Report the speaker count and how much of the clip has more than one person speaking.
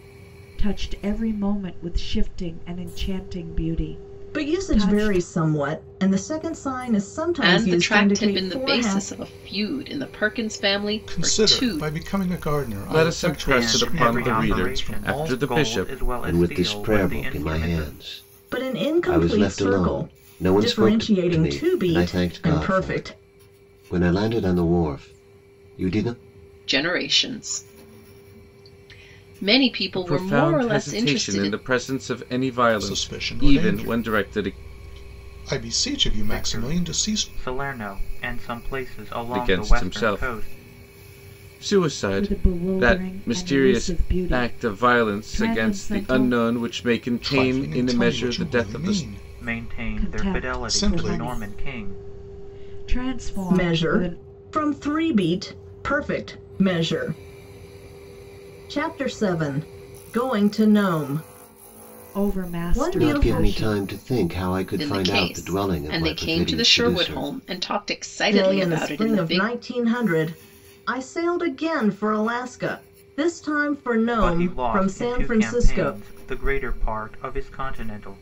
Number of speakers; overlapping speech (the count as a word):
seven, about 45%